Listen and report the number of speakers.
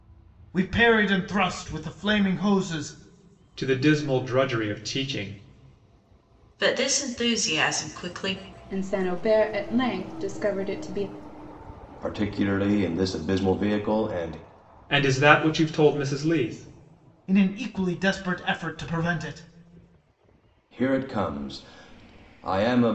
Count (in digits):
5